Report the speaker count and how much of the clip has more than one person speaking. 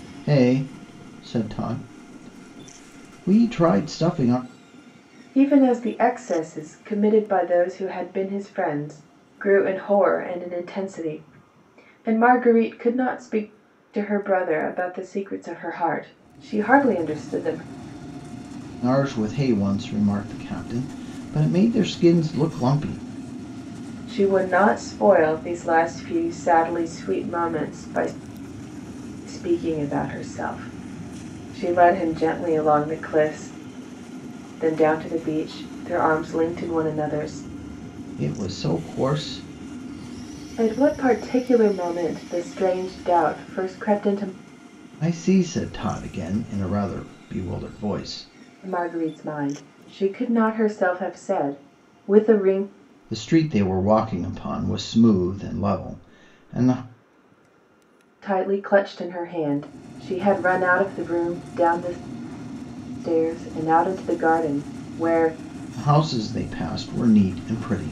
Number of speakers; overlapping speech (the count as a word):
two, no overlap